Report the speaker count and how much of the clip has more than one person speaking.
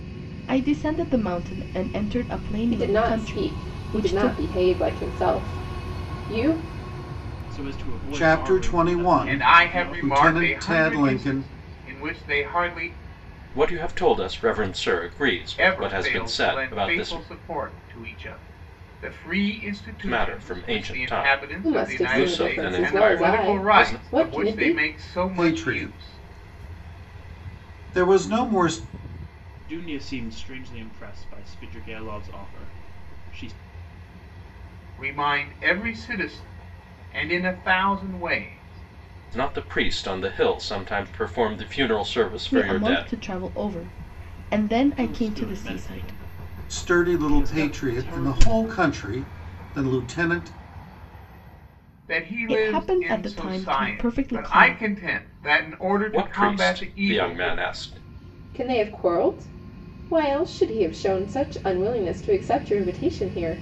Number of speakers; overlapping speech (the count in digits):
6, about 32%